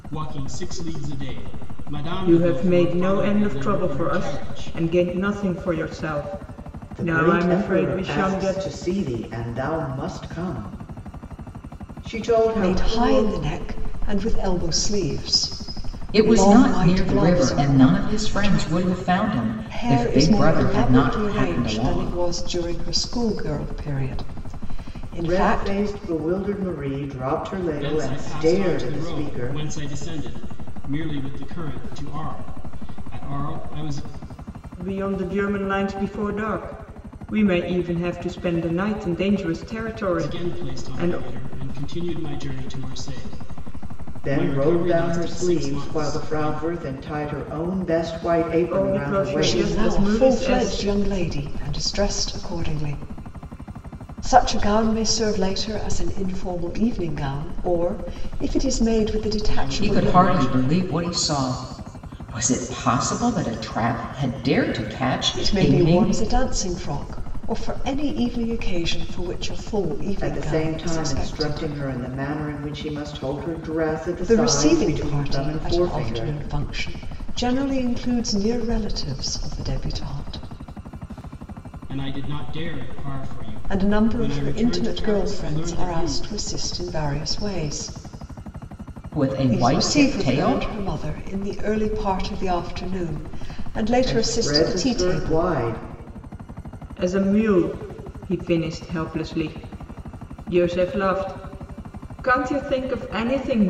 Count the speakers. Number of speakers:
5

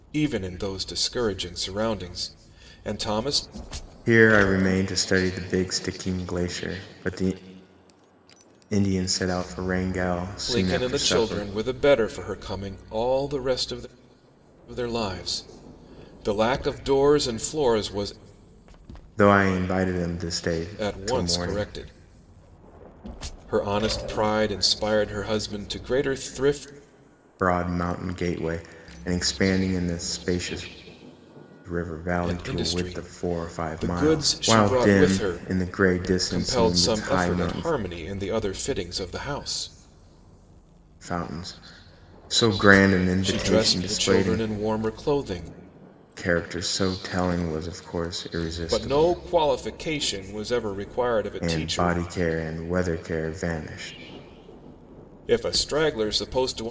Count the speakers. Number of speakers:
2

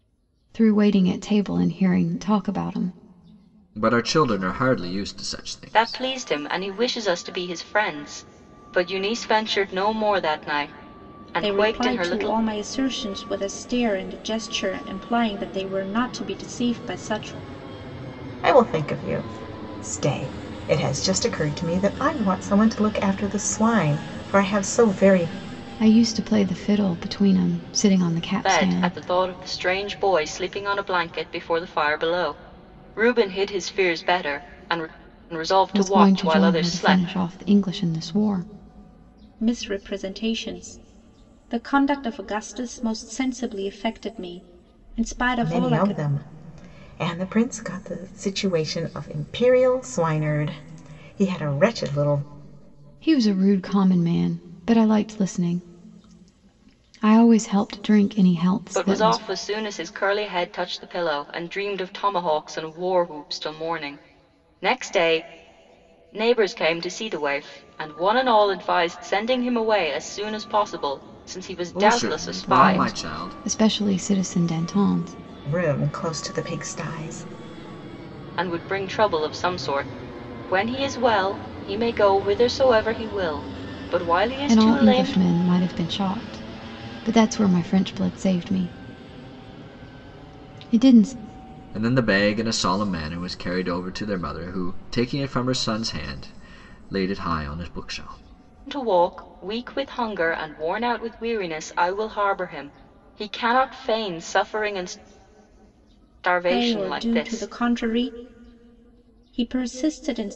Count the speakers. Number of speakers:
5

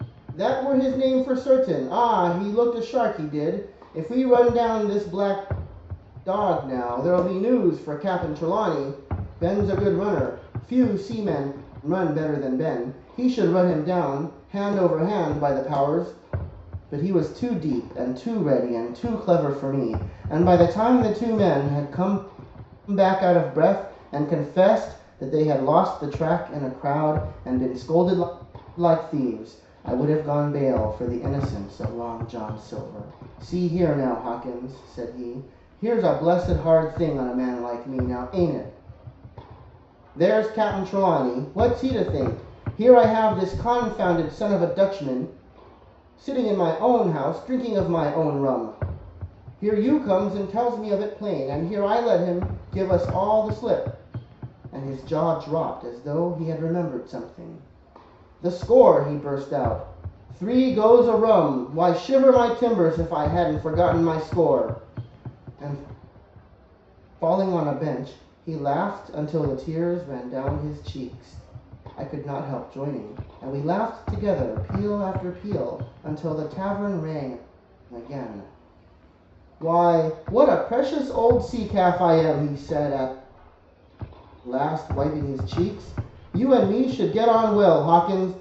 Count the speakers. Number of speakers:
1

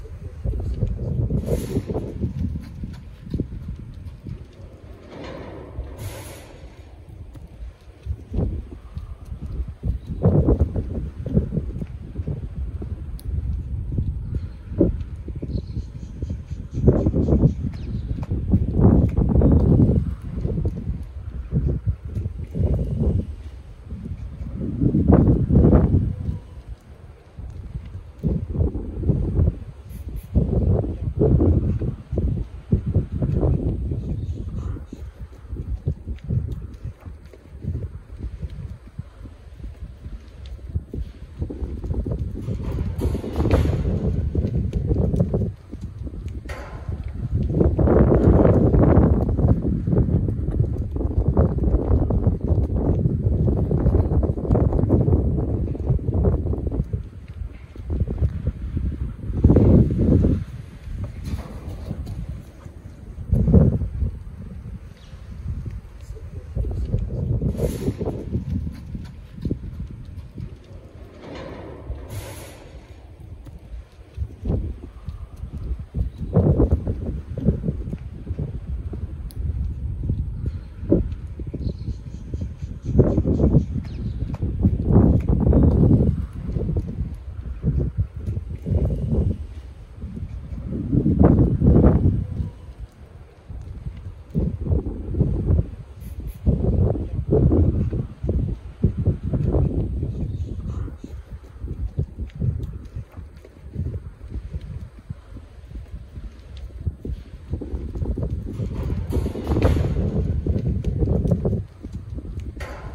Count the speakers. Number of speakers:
0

